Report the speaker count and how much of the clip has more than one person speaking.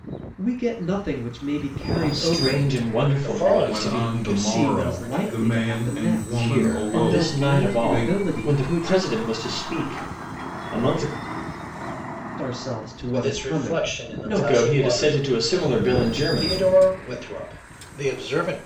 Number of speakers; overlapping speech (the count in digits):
4, about 56%